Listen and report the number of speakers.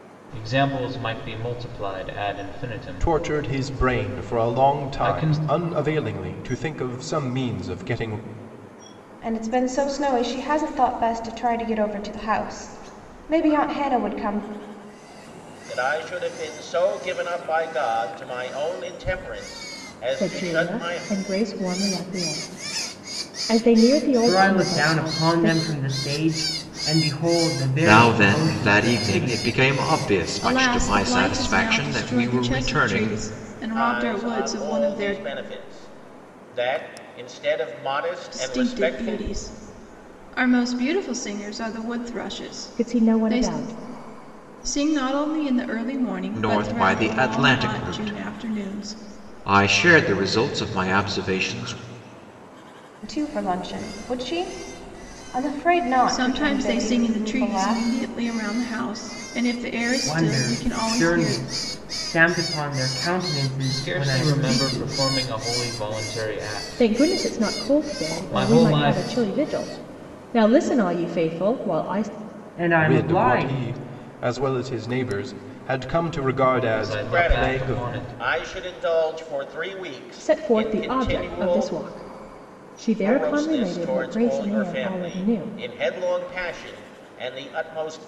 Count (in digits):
8